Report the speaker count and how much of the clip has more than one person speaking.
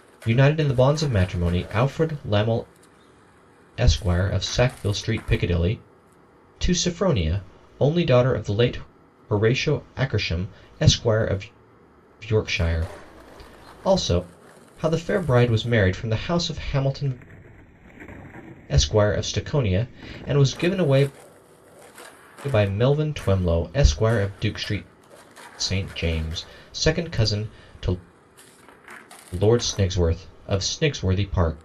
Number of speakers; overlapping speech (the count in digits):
1, no overlap